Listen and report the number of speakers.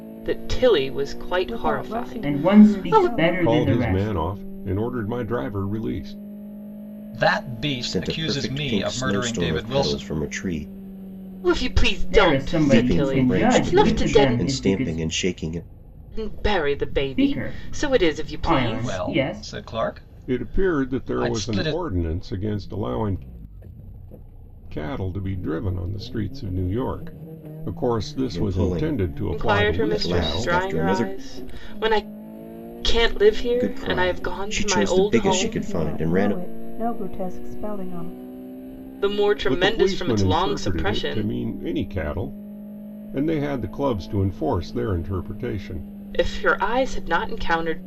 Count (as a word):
six